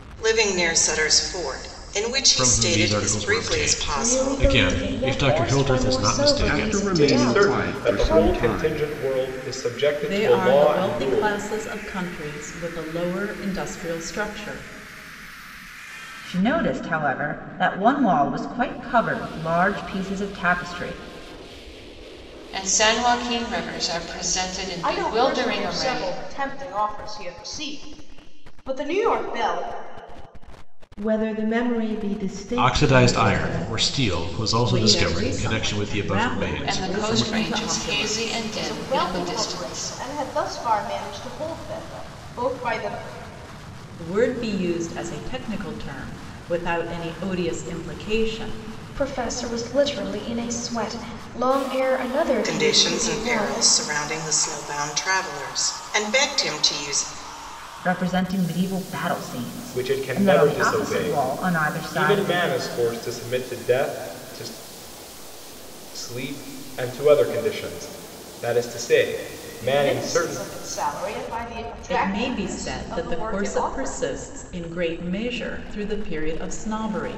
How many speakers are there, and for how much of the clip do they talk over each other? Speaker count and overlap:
ten, about 31%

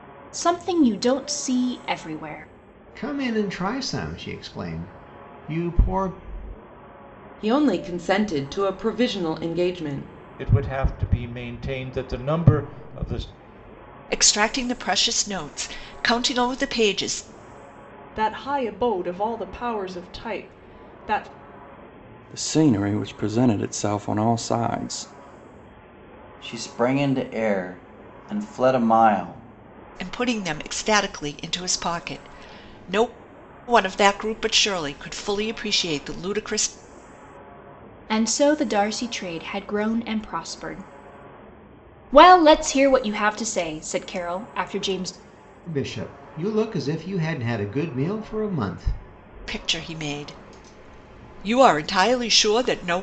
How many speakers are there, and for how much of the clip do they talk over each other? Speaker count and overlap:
eight, no overlap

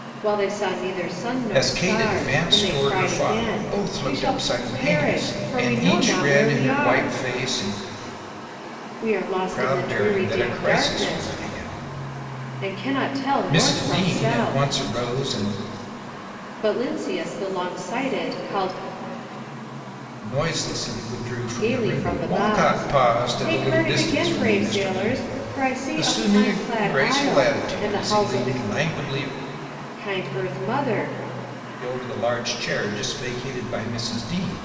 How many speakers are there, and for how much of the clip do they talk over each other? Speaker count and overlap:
two, about 45%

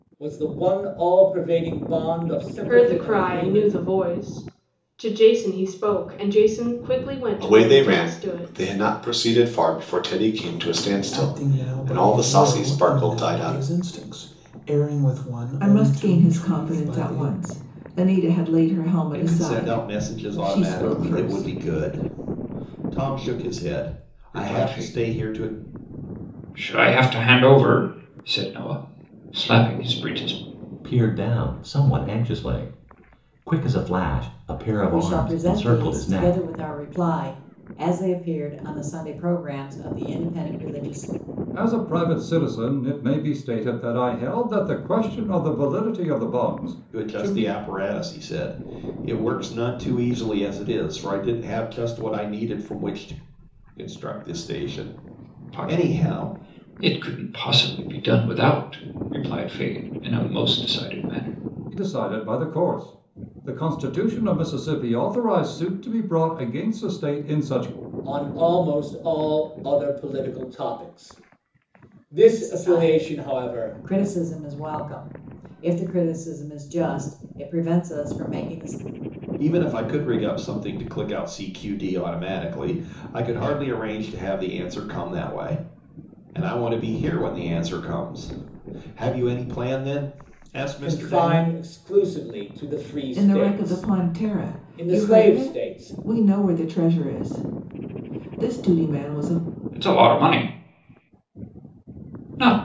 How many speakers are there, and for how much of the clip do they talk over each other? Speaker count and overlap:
ten, about 18%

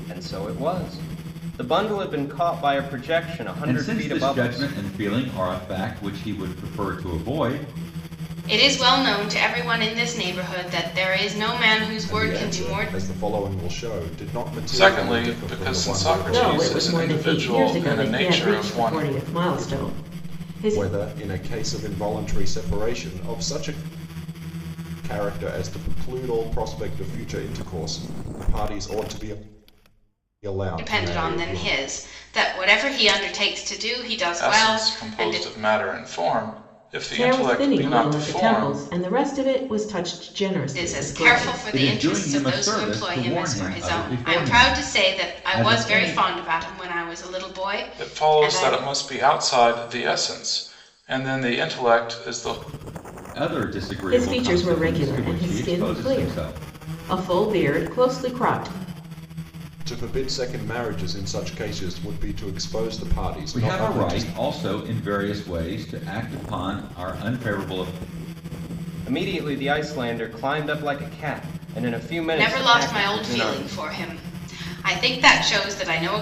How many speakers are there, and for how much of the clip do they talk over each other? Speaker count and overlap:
six, about 30%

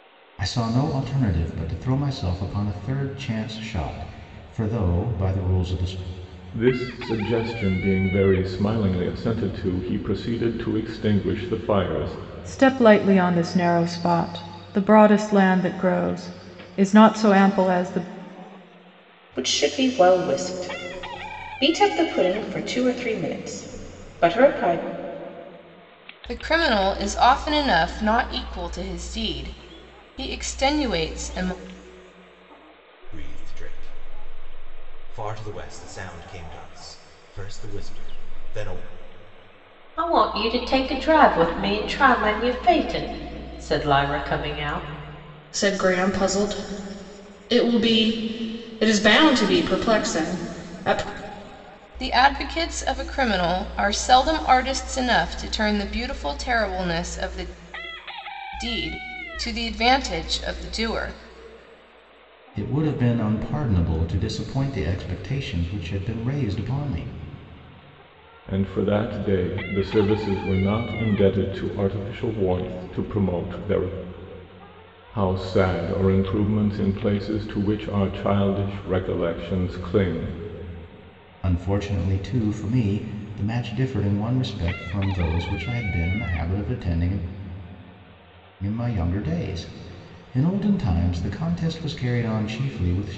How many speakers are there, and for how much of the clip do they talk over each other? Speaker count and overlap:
eight, no overlap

